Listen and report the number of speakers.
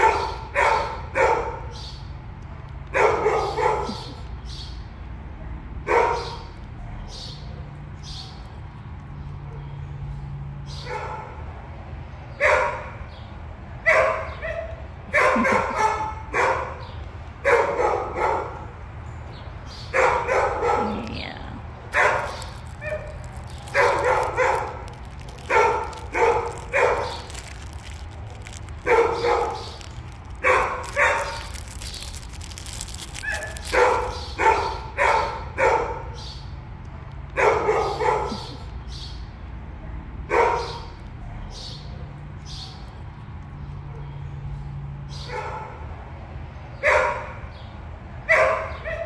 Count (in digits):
0